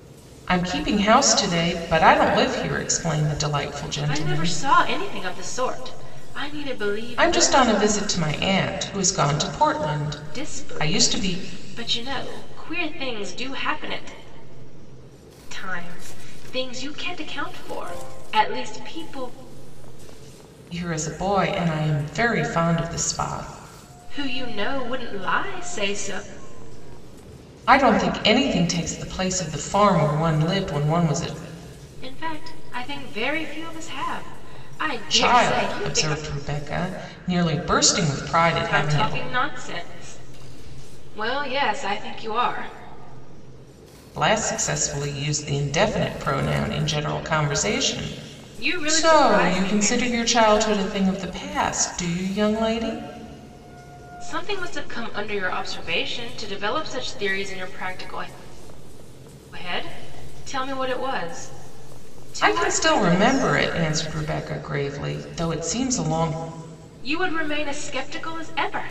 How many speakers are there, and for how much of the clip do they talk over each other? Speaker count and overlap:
2, about 9%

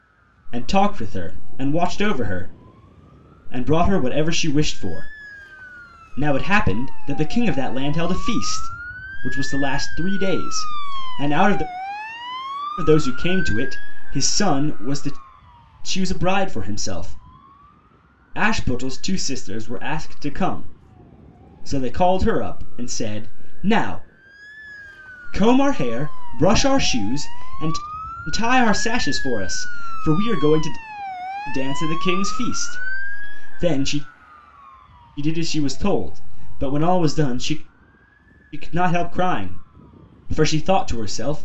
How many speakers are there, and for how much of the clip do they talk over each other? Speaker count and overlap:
1, no overlap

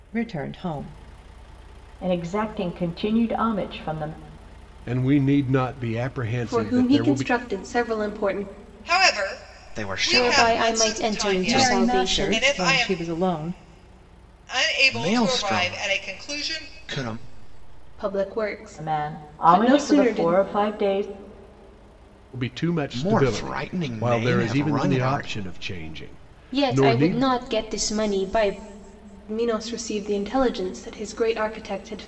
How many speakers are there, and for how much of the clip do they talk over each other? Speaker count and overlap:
7, about 33%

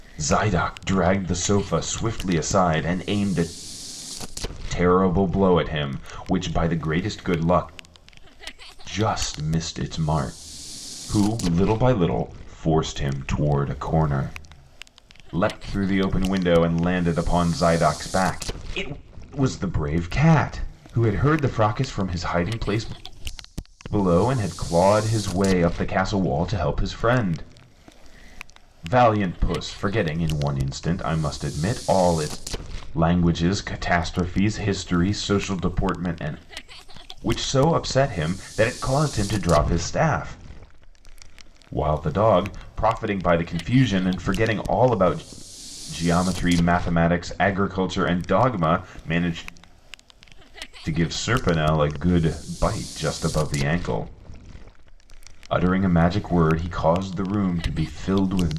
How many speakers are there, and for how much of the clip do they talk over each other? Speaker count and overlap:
1, no overlap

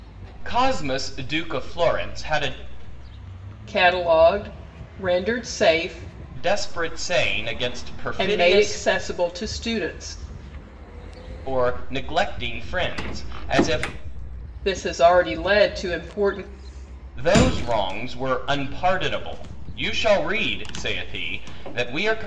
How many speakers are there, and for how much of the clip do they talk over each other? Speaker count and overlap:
2, about 3%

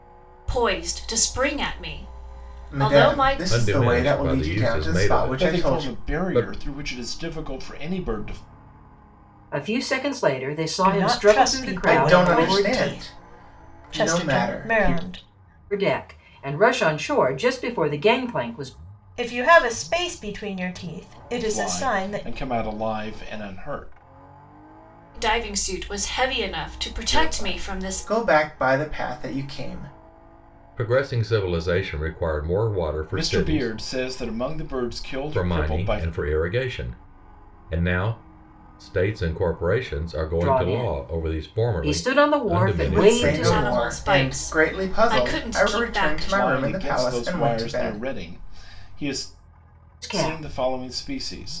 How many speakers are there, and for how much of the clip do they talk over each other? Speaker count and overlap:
6, about 36%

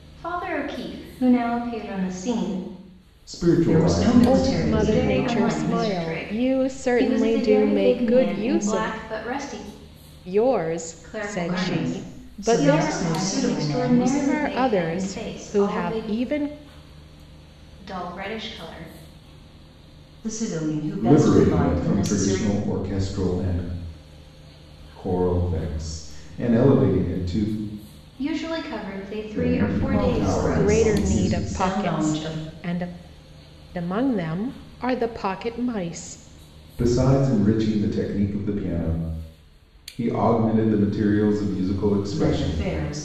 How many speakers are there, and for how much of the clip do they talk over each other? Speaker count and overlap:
4, about 36%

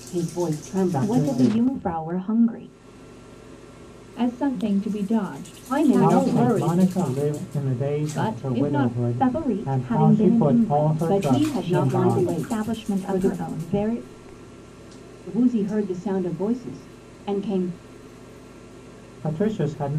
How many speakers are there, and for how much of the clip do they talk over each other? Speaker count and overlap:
4, about 42%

